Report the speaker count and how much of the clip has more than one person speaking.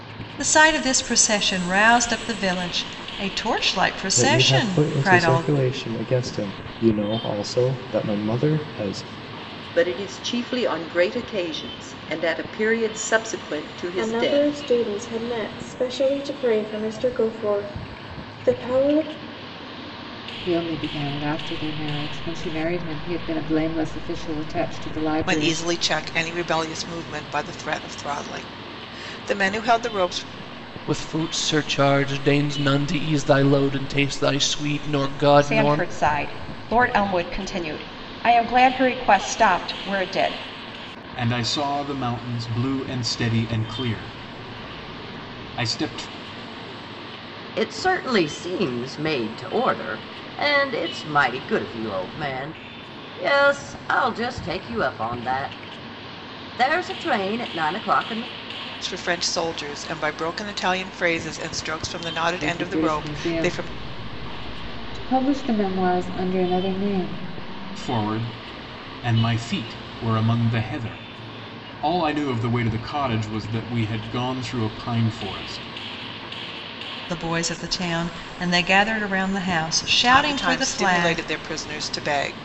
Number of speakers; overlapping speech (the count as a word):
ten, about 7%